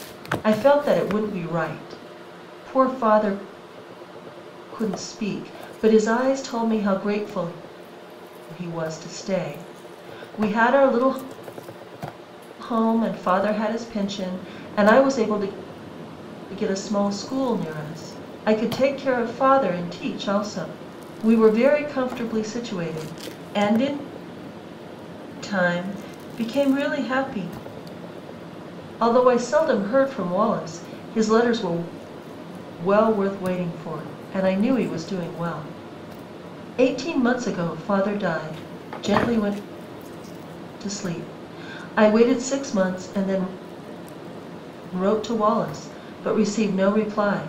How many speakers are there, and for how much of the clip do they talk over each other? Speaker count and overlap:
one, no overlap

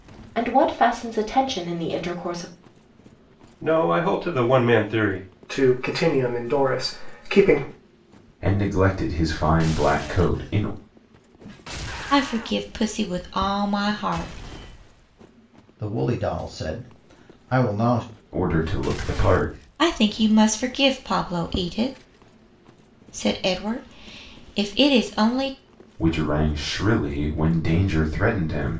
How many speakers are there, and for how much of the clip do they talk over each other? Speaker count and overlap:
six, no overlap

